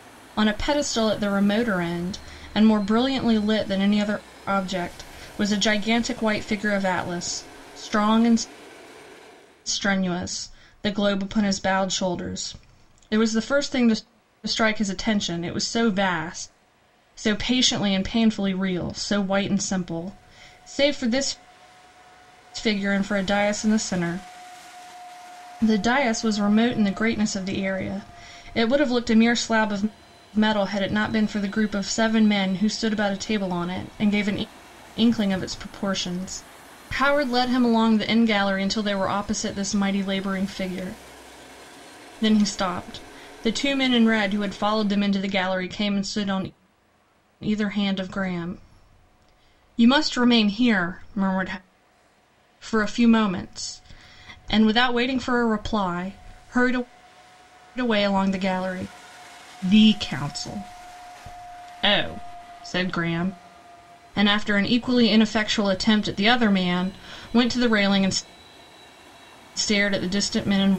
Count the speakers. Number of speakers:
1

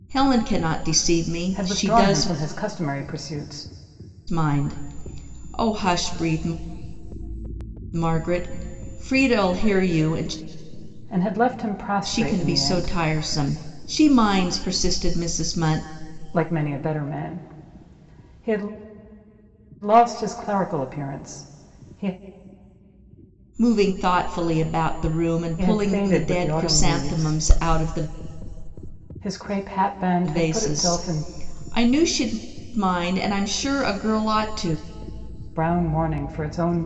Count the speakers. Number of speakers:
2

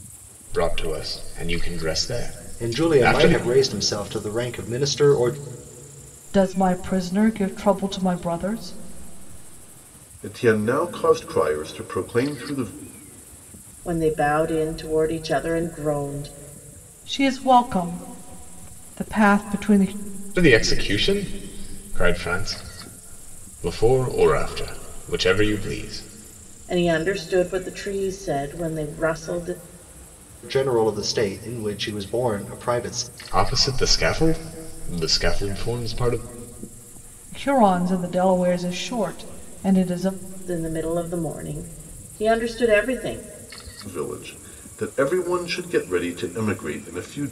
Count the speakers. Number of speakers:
5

